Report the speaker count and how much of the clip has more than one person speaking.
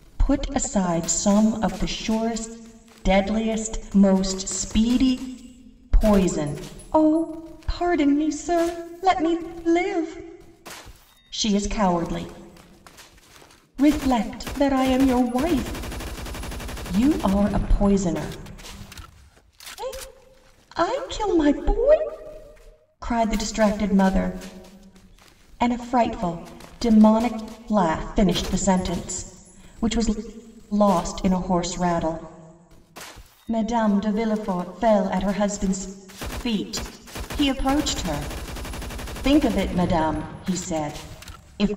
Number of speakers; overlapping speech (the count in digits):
1, no overlap